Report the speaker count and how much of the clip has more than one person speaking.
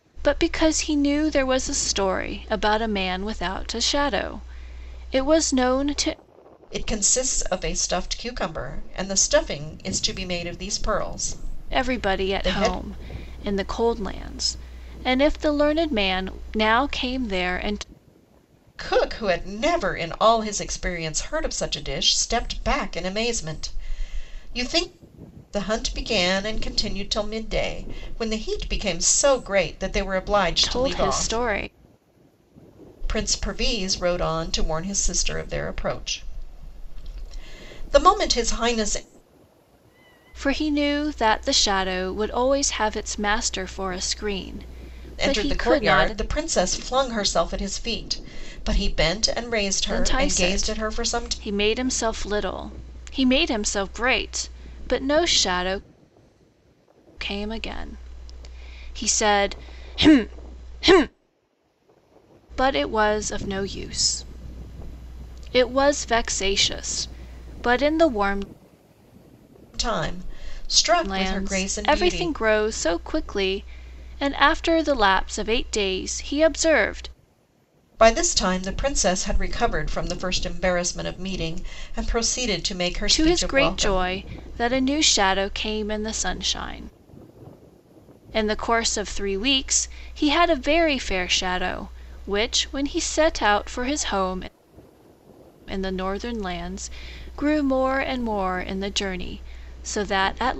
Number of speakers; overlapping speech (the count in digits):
2, about 7%